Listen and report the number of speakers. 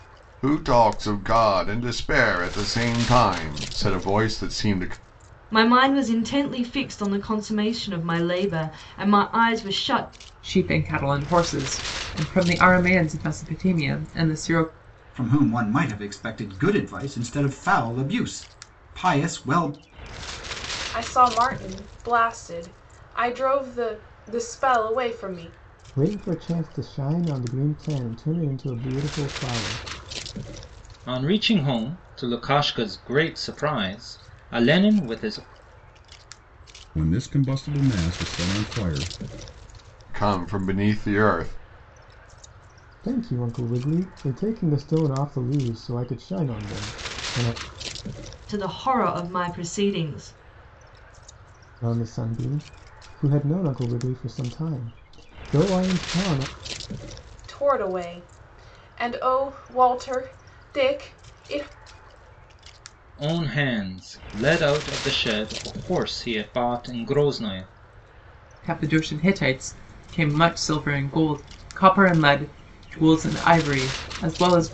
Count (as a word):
eight